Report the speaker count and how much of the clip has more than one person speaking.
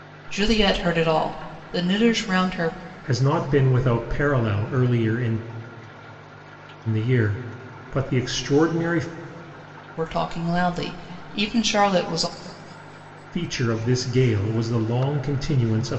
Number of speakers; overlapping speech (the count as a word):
two, no overlap